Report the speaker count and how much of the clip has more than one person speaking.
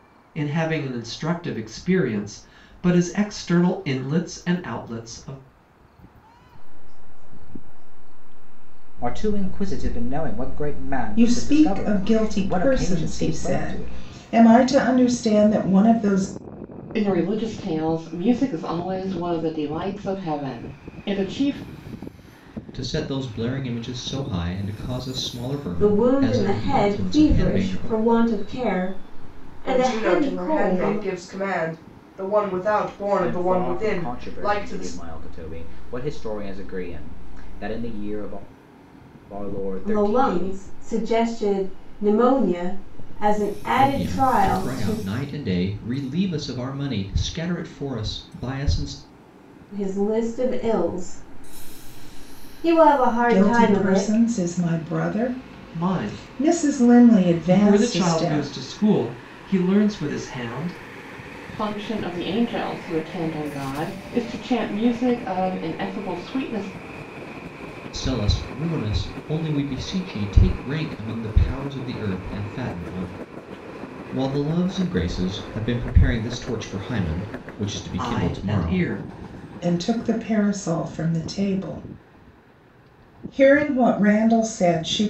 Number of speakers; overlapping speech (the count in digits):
8, about 20%